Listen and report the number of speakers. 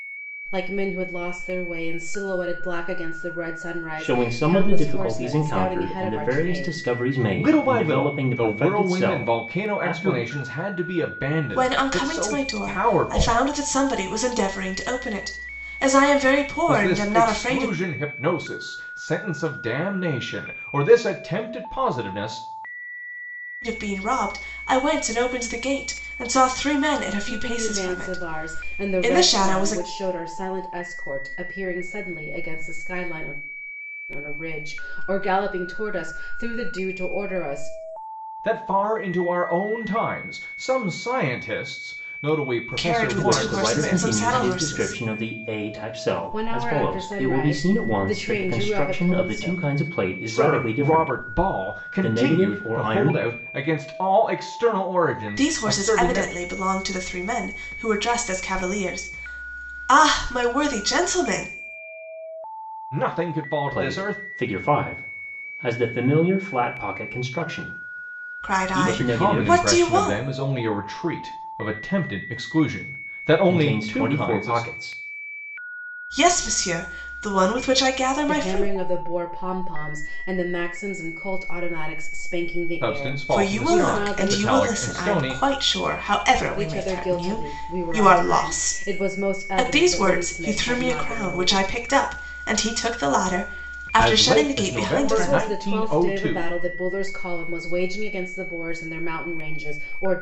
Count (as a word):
four